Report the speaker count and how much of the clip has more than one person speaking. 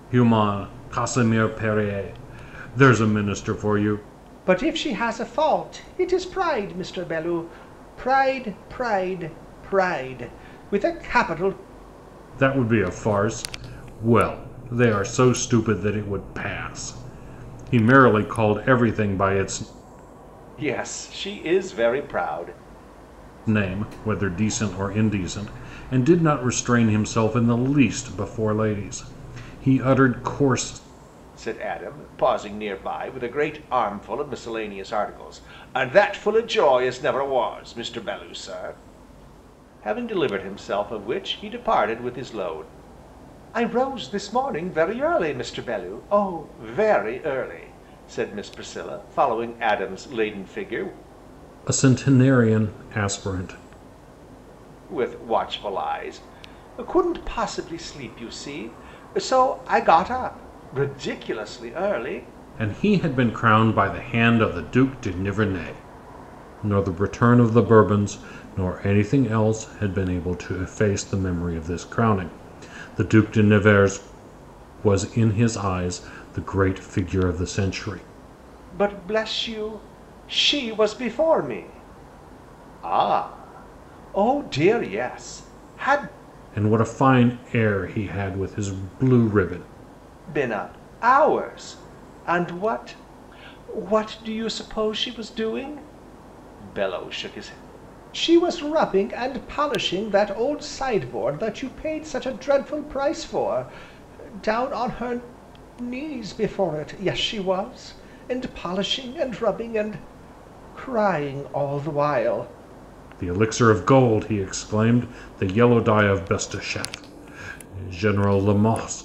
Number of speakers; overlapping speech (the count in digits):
2, no overlap